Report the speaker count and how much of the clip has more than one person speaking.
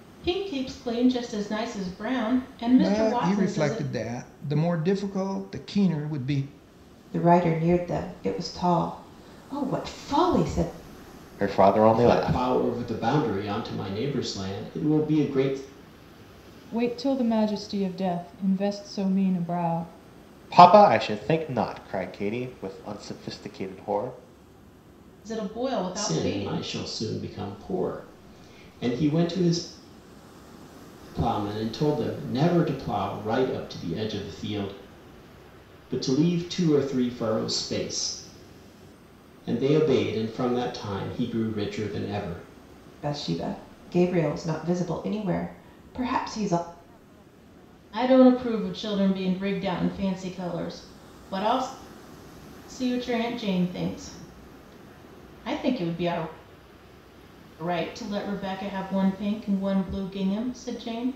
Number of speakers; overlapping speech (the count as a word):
six, about 4%